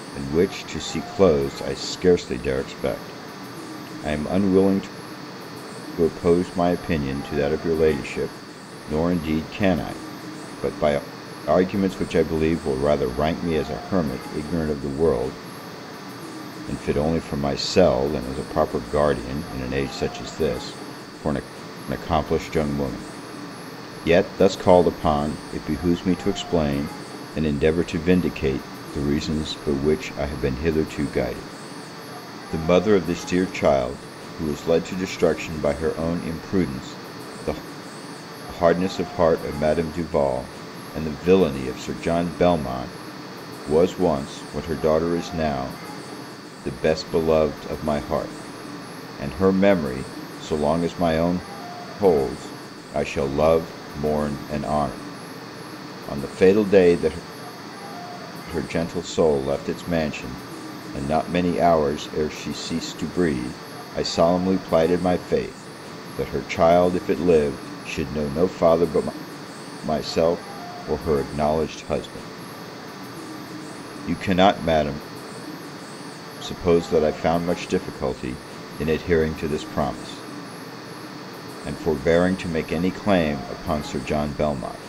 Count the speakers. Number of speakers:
1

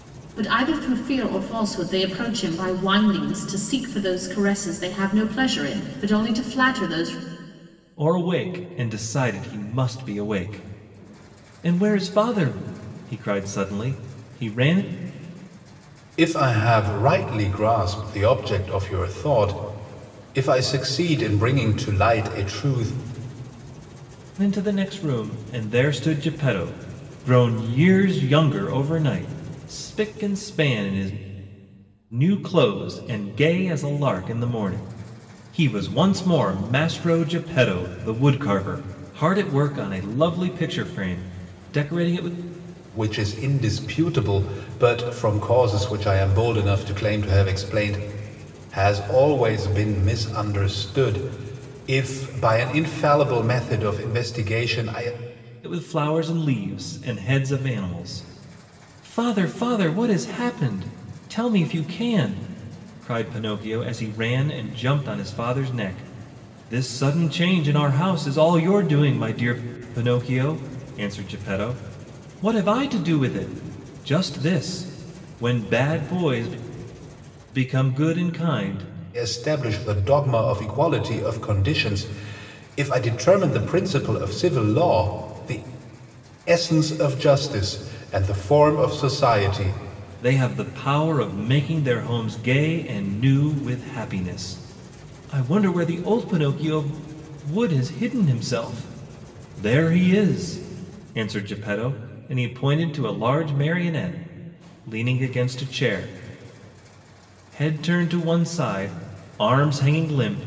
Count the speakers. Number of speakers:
3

